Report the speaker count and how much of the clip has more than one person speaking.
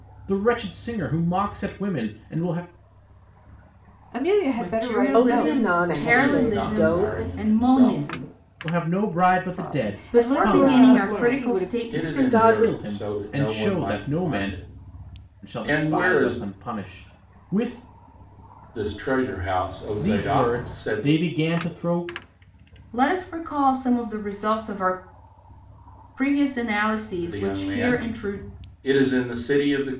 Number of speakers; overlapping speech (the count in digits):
5, about 40%